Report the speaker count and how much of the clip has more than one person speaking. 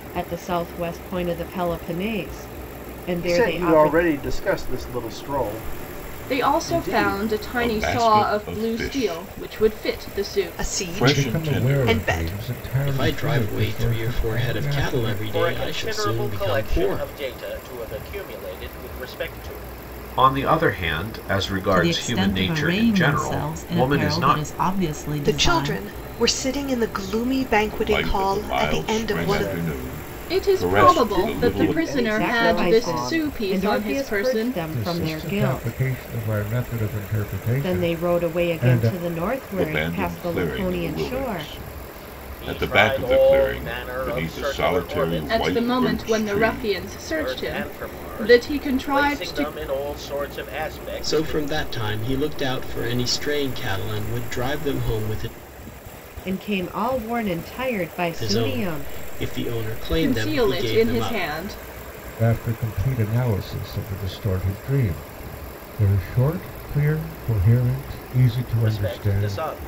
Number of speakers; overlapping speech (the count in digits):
10, about 53%